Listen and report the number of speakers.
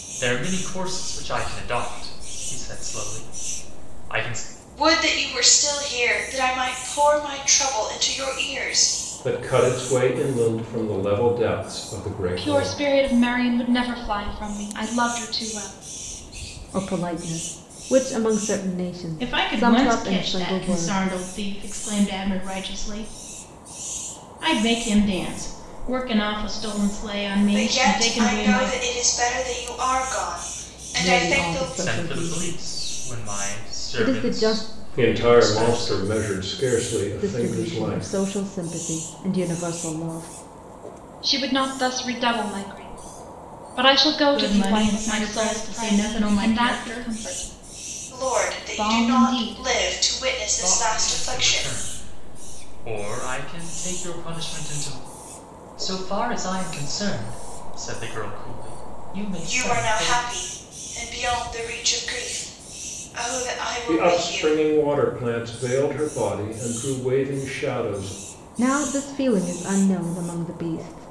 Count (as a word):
six